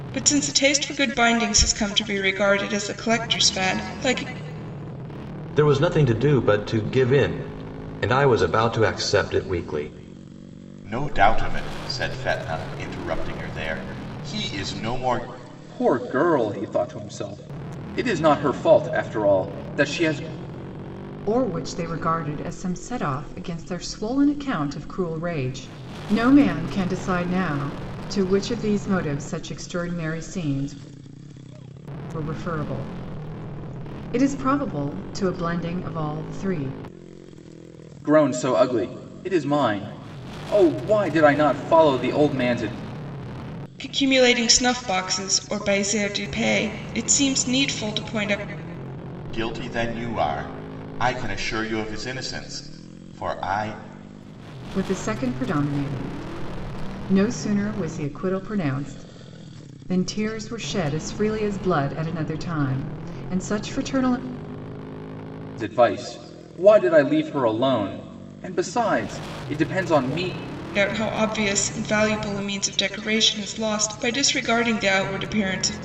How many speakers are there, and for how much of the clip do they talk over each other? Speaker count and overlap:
5, no overlap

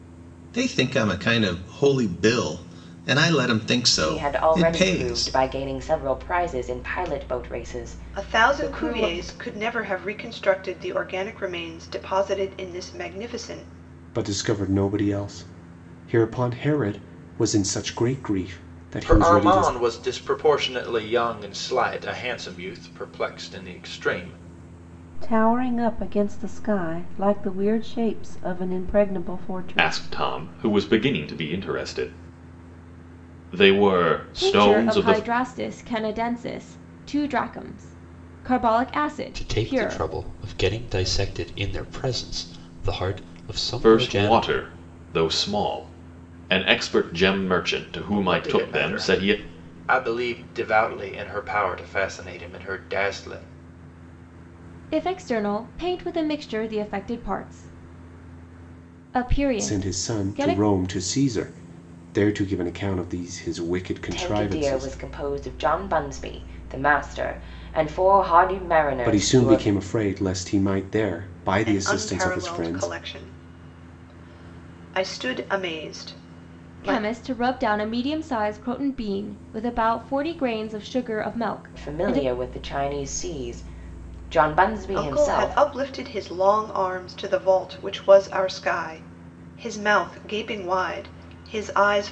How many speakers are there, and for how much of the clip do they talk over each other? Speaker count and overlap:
9, about 14%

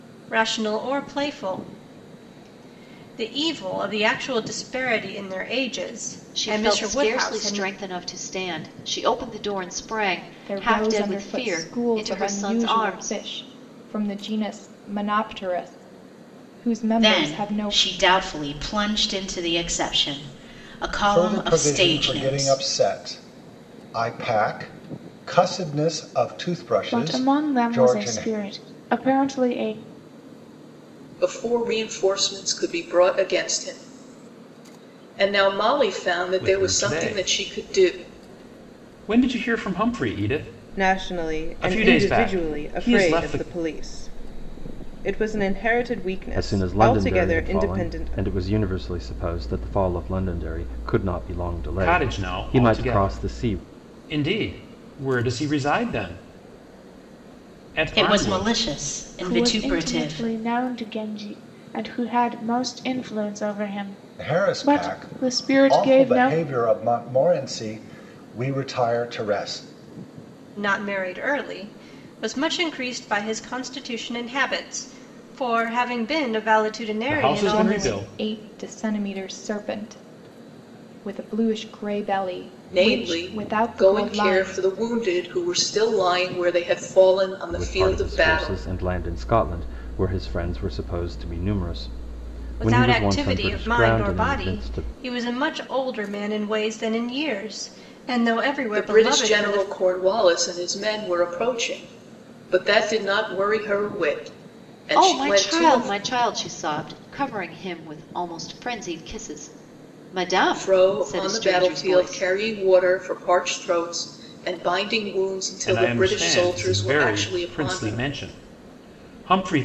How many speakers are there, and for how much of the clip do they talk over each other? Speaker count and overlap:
10, about 28%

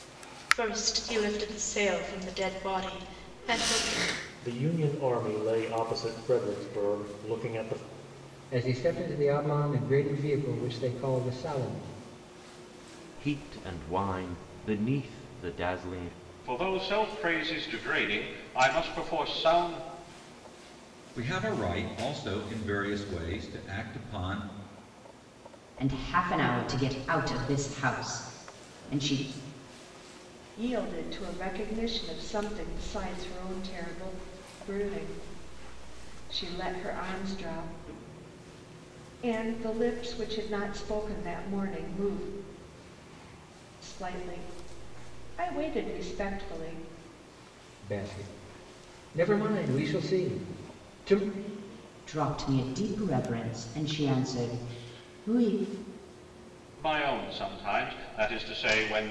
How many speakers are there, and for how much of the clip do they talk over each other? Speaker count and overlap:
8, no overlap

